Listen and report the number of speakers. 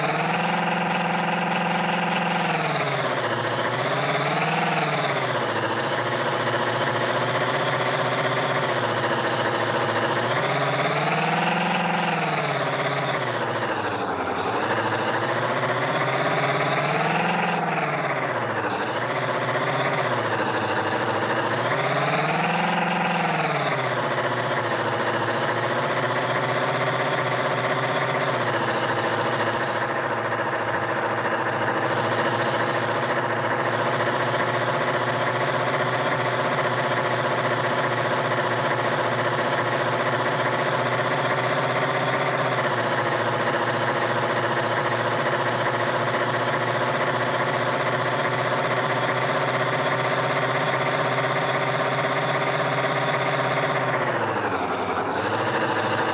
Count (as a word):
zero